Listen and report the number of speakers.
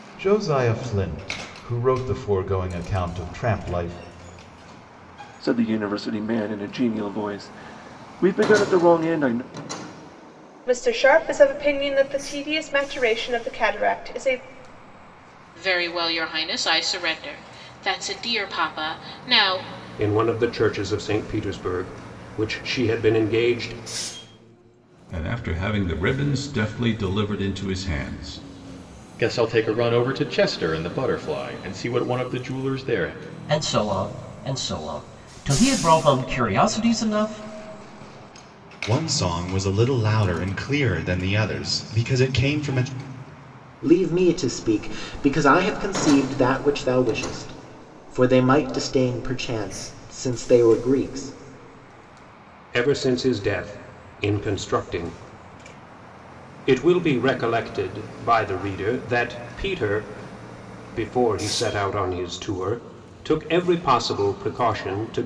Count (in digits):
10